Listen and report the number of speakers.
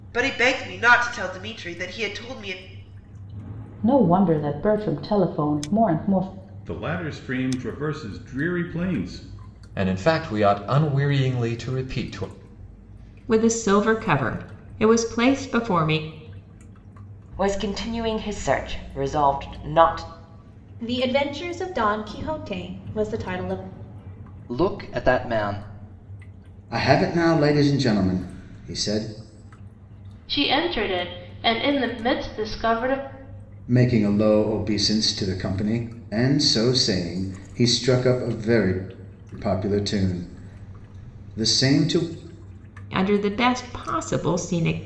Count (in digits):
10